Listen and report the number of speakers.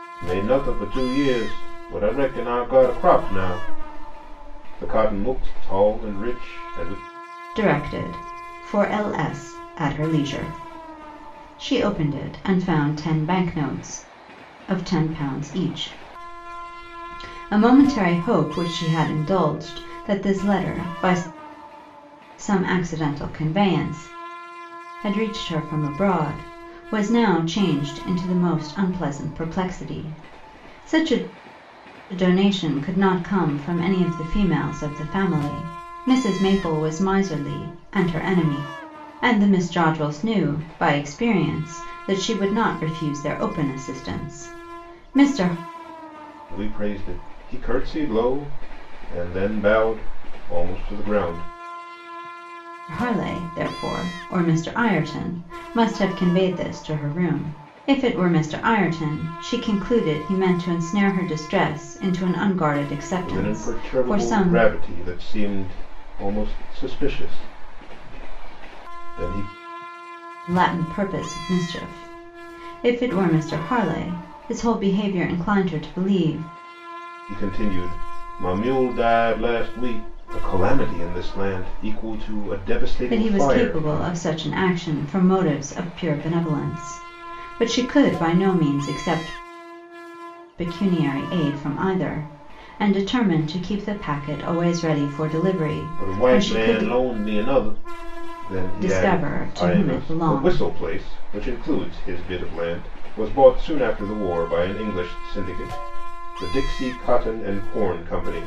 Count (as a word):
two